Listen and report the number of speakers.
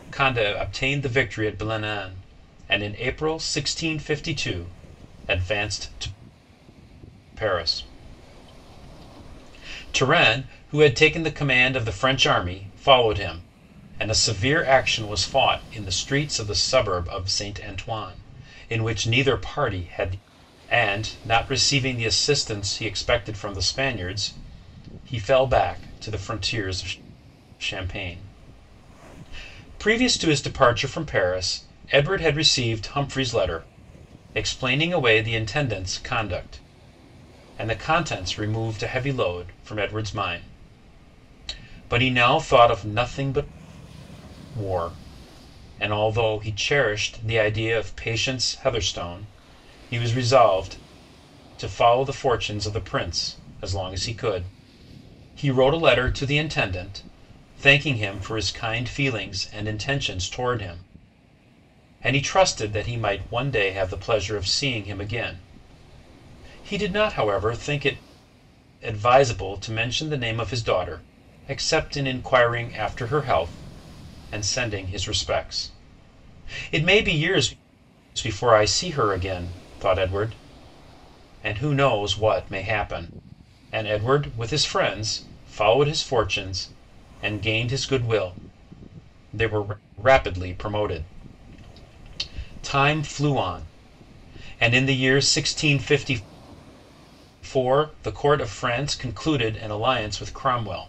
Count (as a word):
one